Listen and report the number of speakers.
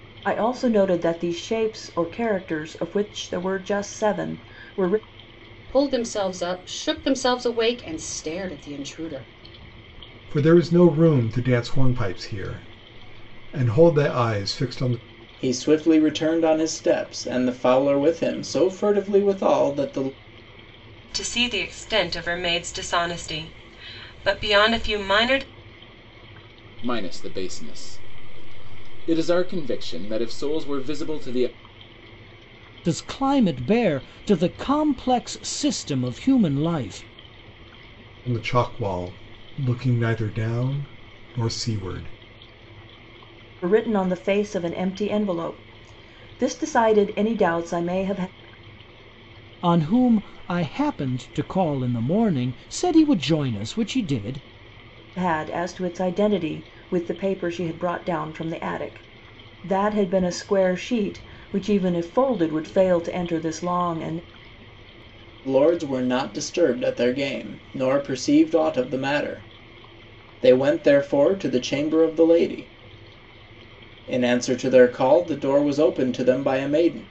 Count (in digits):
7